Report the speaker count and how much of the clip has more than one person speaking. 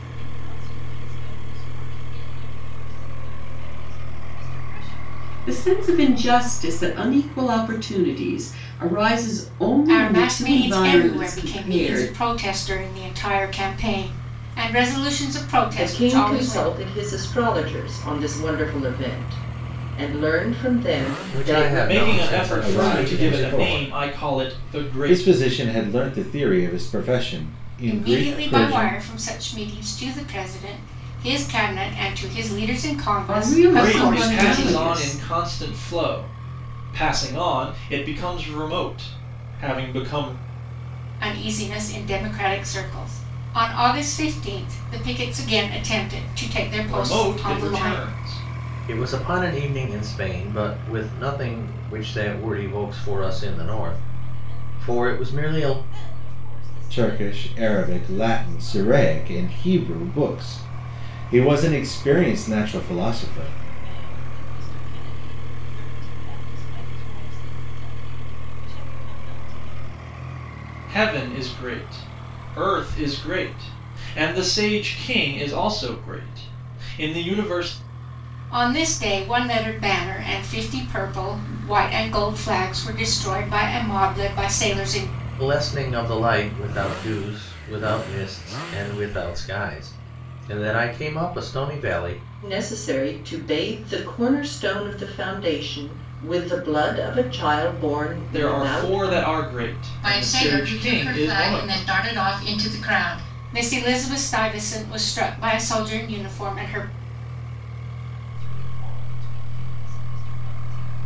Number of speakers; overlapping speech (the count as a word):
seven, about 20%